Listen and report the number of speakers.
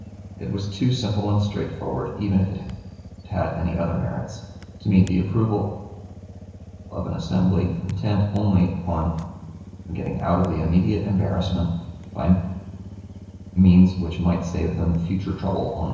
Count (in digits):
1